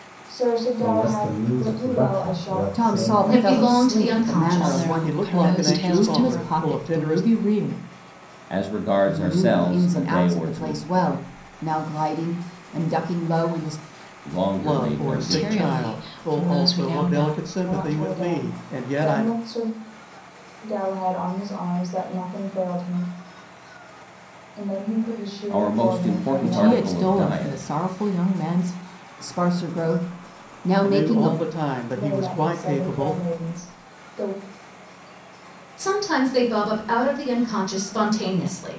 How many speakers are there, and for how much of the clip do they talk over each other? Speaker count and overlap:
eight, about 43%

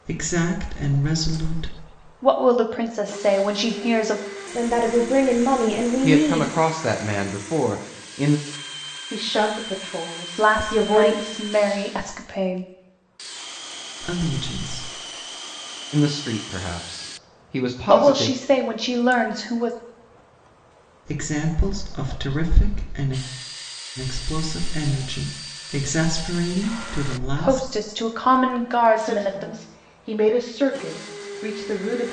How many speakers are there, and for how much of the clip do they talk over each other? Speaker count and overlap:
five, about 10%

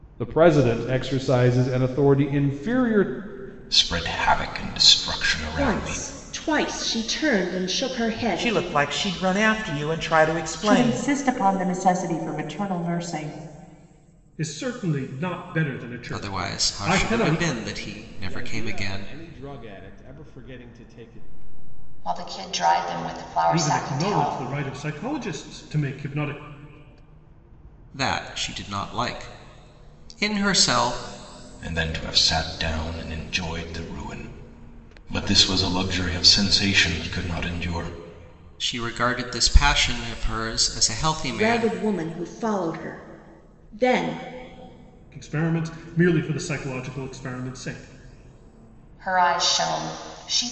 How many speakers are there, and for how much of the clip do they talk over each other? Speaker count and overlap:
nine, about 10%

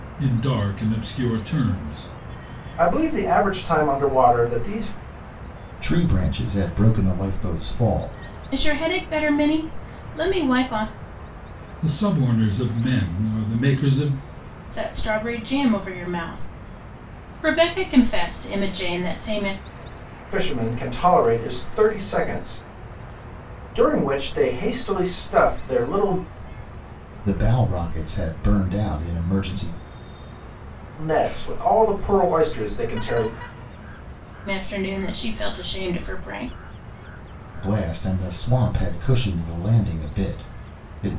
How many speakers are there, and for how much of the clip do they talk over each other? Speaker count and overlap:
four, no overlap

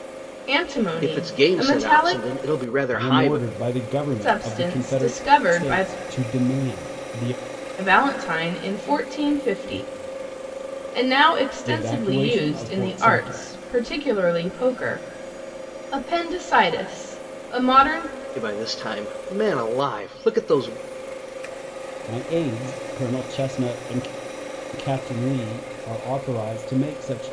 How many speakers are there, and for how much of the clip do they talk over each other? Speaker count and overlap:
three, about 19%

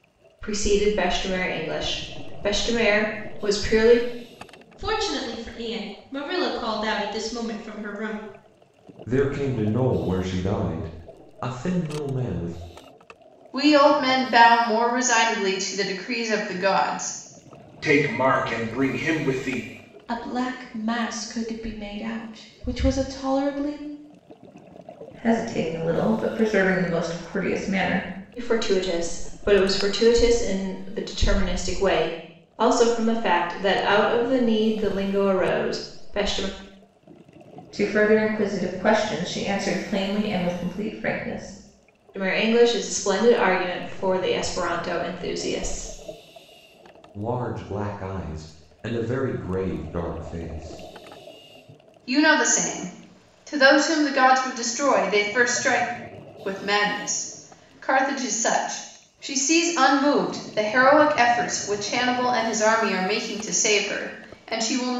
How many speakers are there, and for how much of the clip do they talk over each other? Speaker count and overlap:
seven, no overlap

